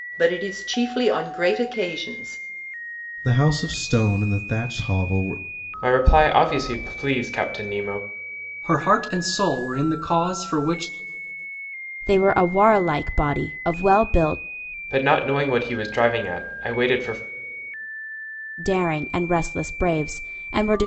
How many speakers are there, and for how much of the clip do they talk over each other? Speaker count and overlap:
5, no overlap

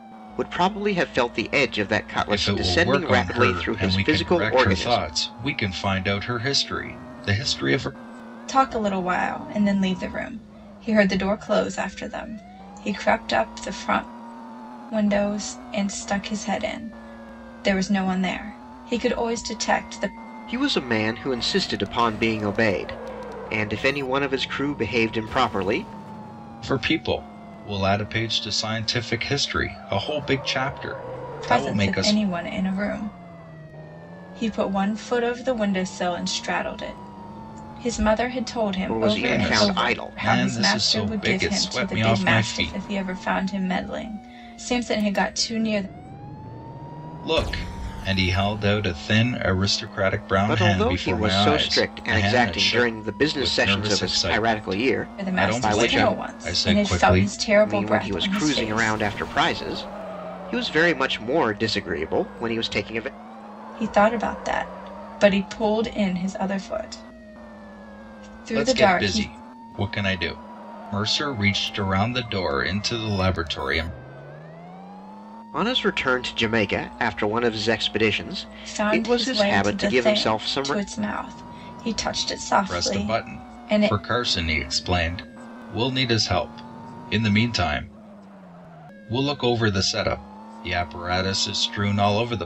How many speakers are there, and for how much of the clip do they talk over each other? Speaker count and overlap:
3, about 22%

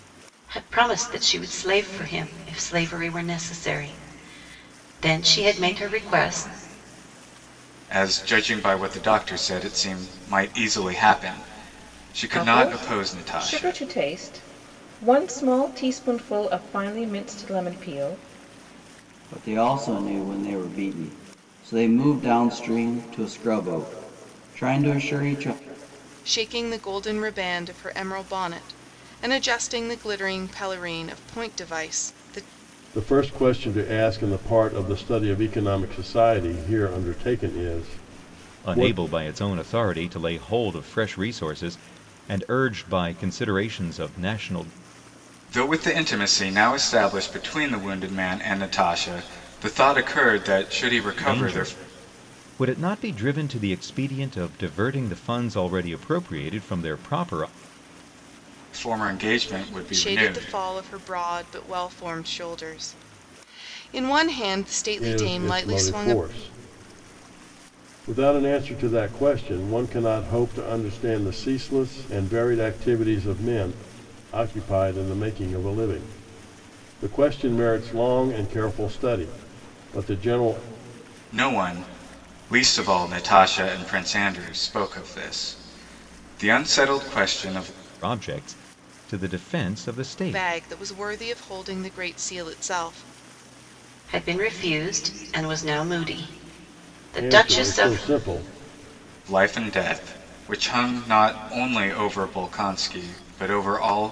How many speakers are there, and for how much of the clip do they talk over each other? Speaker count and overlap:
7, about 5%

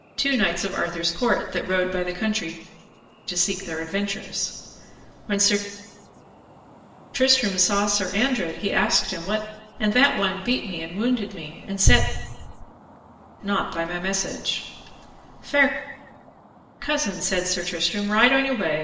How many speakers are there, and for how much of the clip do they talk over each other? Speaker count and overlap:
1, no overlap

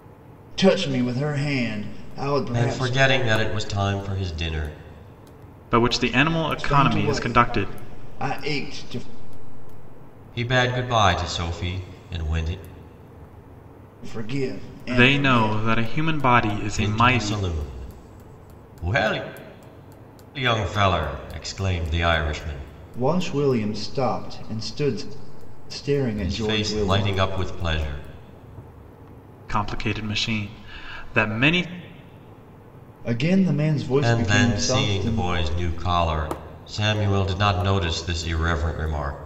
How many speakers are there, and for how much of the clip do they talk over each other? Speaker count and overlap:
3, about 13%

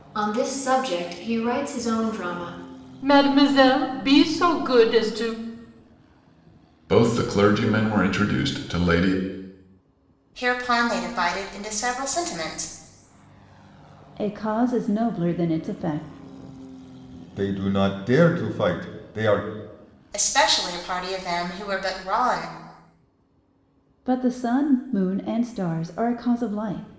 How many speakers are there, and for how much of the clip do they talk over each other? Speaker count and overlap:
6, no overlap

